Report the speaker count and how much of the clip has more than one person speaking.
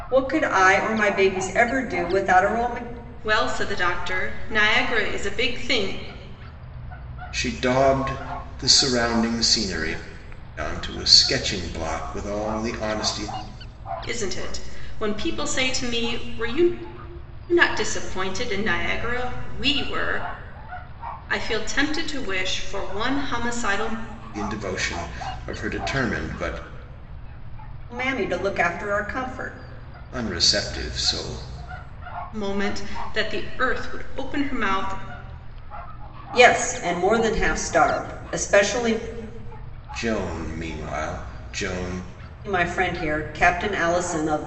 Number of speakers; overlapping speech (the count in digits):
3, no overlap